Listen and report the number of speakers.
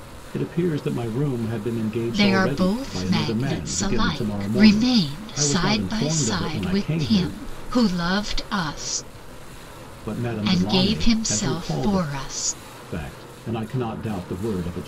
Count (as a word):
two